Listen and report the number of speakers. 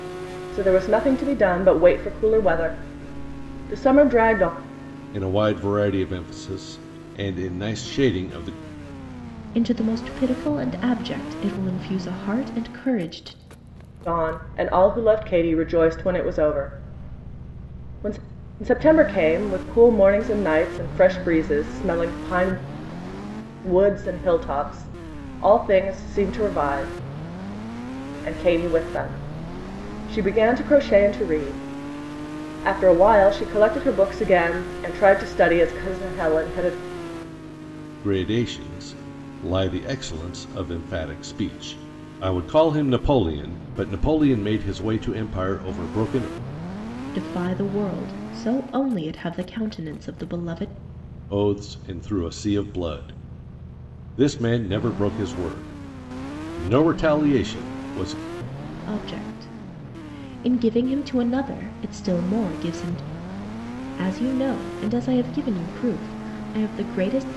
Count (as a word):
three